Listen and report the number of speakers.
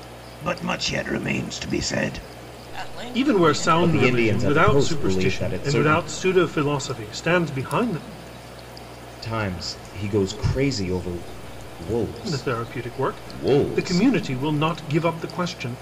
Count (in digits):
4